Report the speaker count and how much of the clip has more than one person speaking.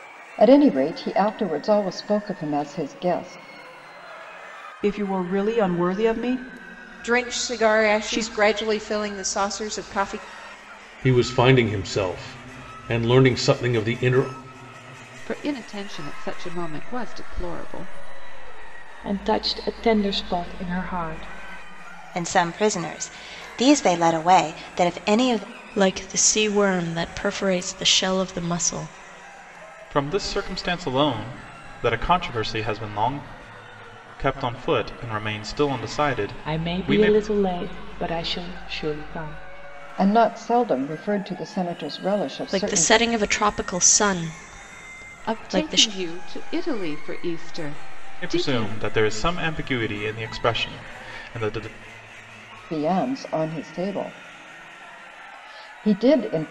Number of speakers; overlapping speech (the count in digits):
9, about 7%